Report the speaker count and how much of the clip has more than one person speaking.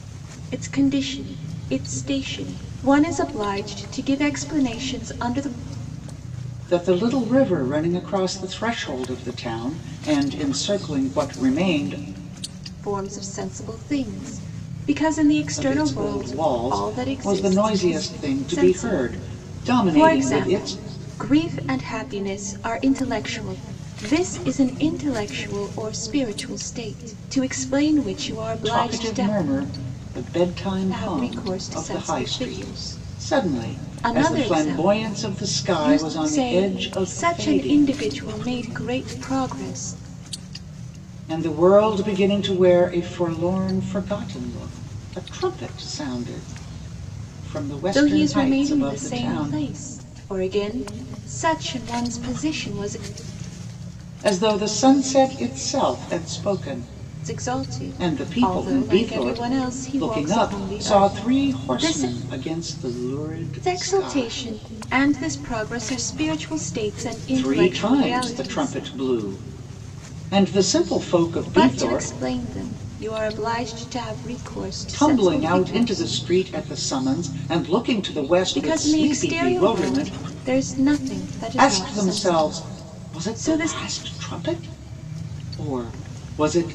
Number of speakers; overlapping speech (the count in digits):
2, about 30%